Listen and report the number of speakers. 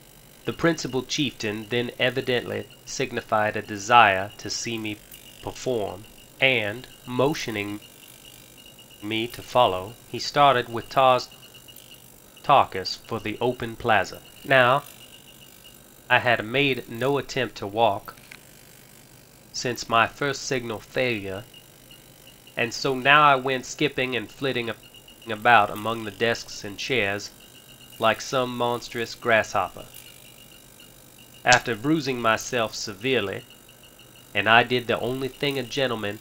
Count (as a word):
one